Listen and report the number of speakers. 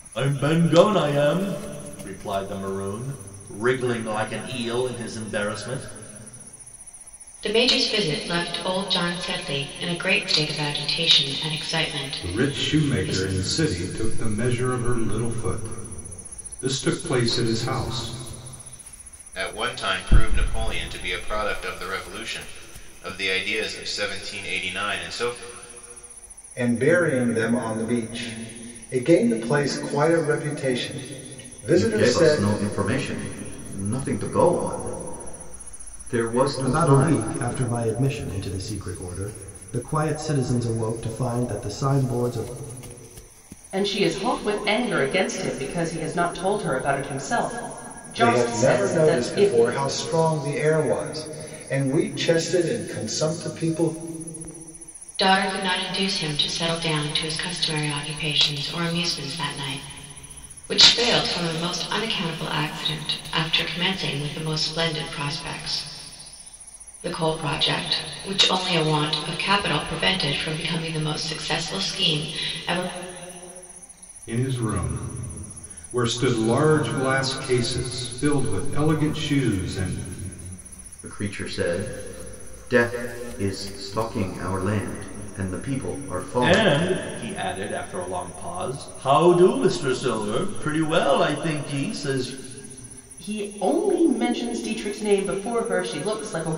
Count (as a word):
eight